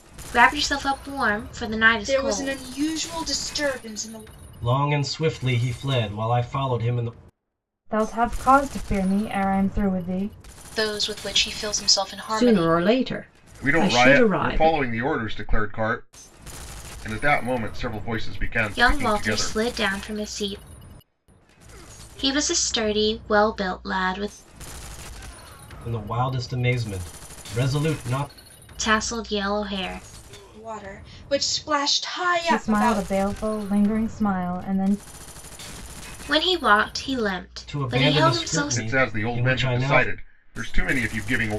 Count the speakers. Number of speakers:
7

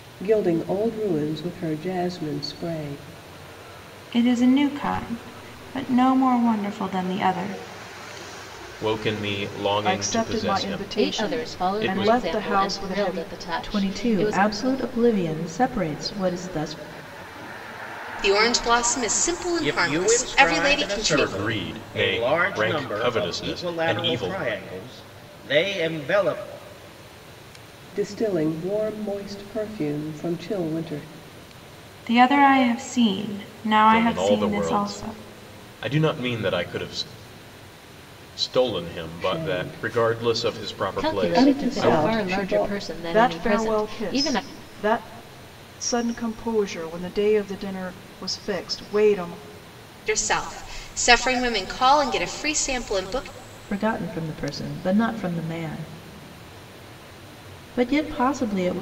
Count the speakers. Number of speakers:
8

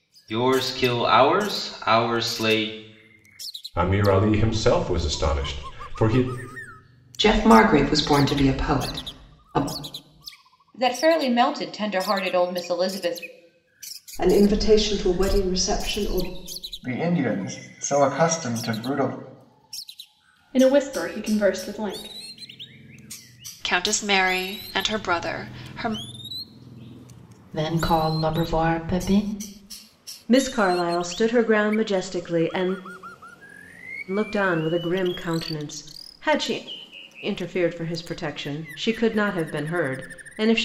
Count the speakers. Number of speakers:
10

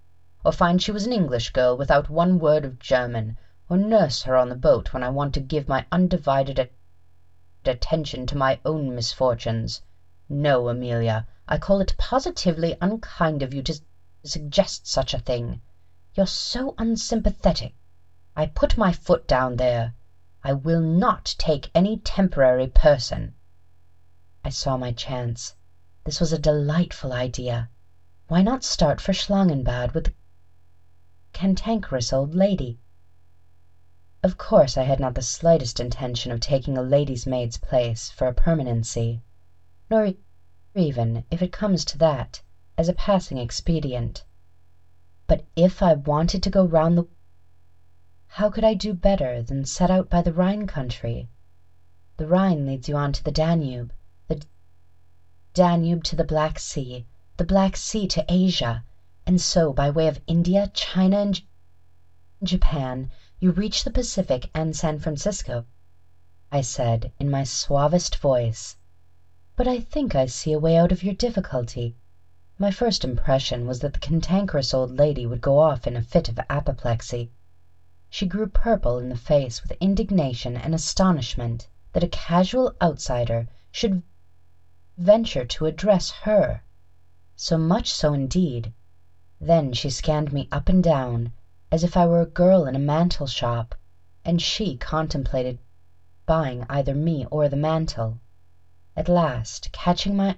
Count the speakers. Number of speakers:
1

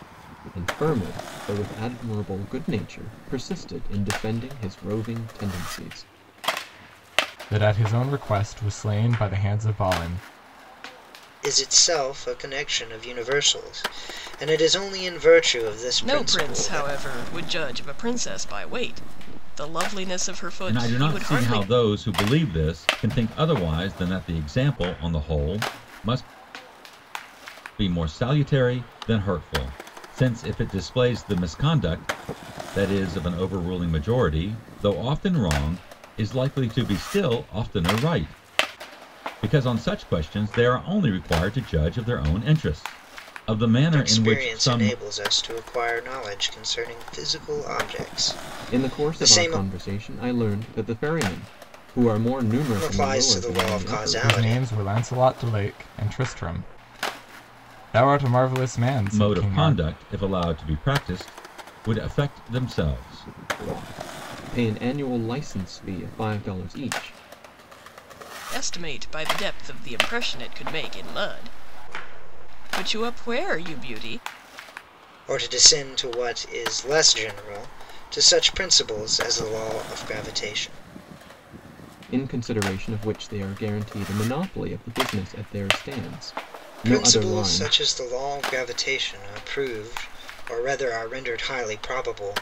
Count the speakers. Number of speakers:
5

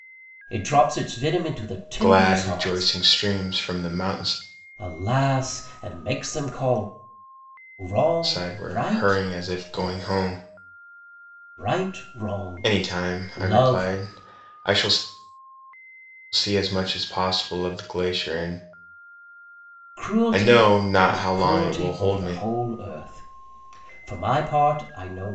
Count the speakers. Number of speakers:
2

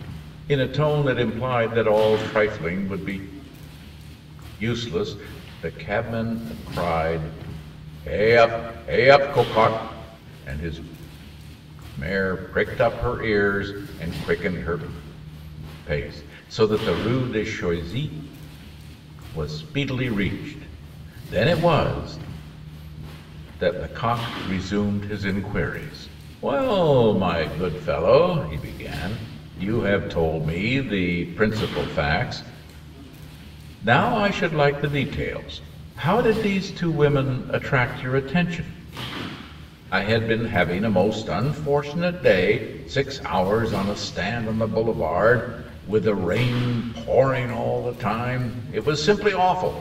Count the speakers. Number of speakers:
1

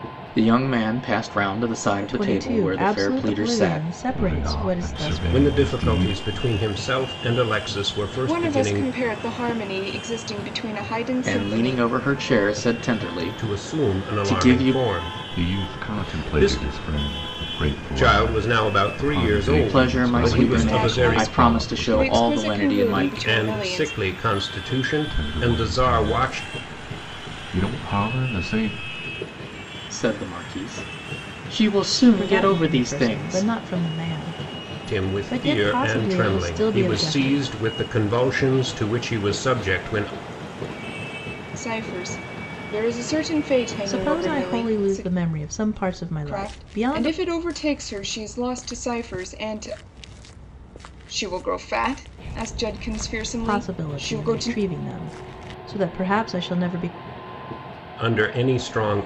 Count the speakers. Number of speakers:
5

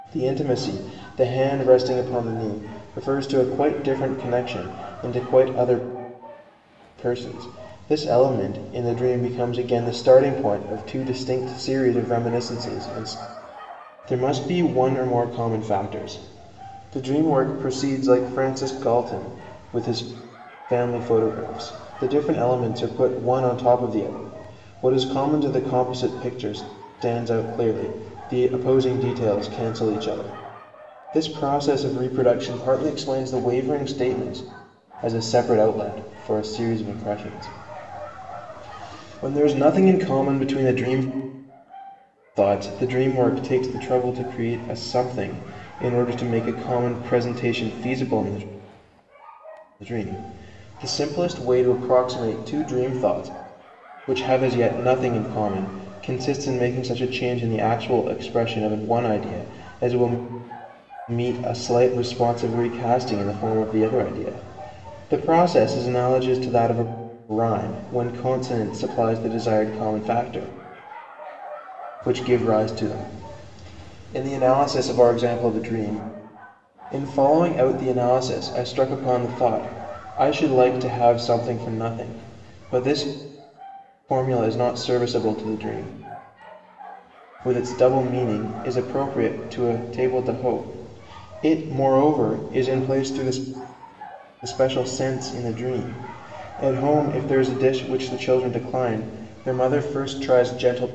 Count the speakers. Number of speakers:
1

